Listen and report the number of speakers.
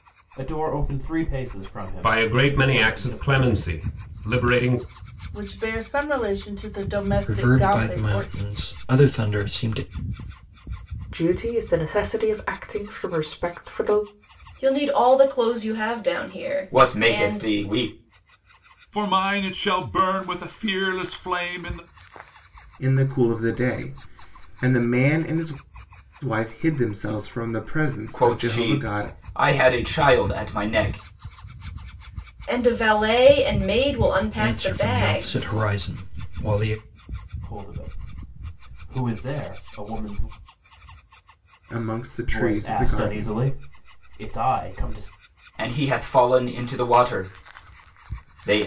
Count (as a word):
nine